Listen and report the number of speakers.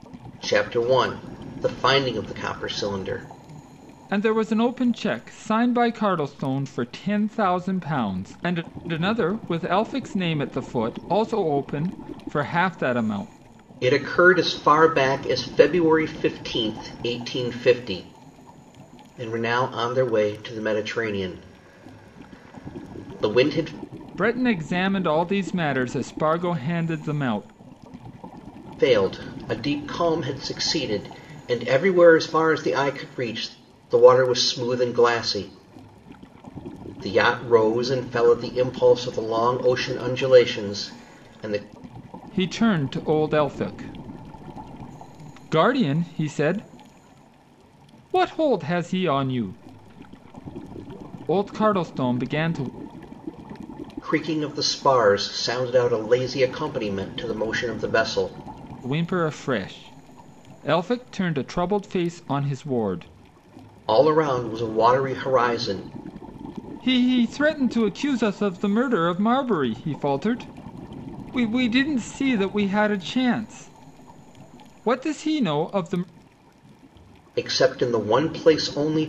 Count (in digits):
2